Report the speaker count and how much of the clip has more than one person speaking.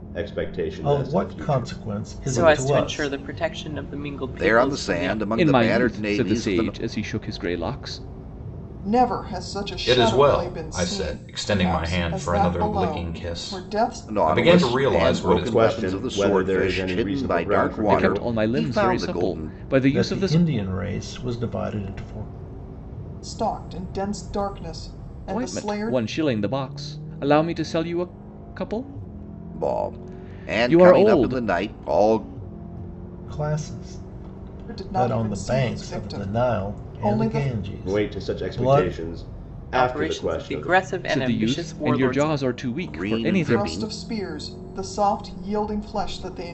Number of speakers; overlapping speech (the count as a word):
seven, about 53%